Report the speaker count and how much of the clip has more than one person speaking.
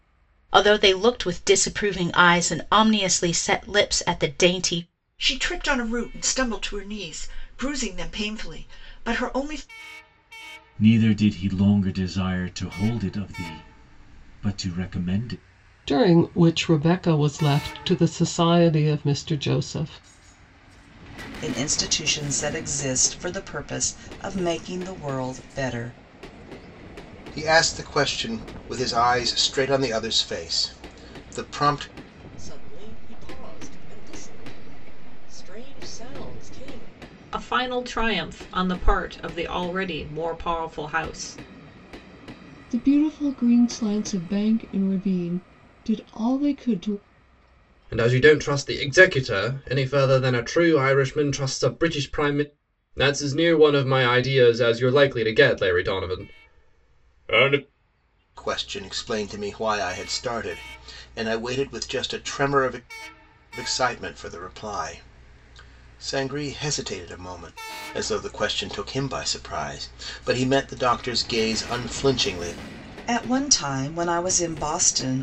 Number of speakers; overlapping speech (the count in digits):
10, no overlap